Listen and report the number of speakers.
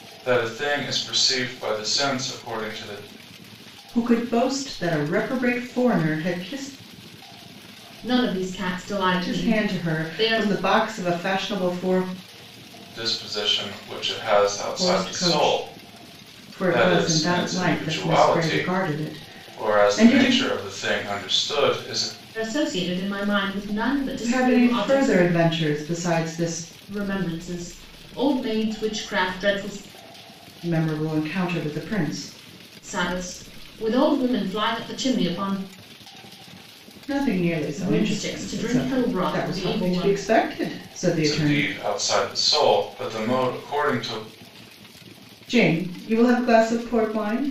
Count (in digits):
3